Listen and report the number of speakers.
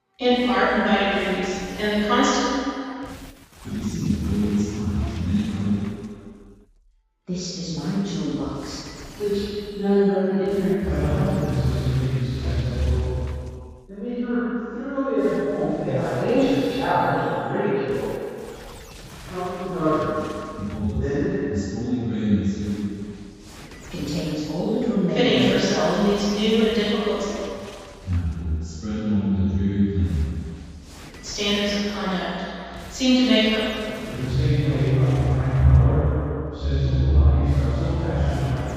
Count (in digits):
7